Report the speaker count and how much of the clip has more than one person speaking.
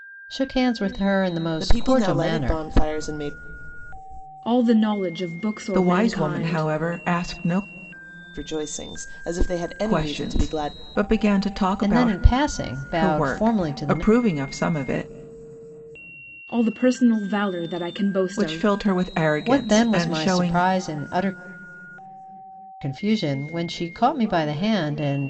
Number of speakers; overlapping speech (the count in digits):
4, about 25%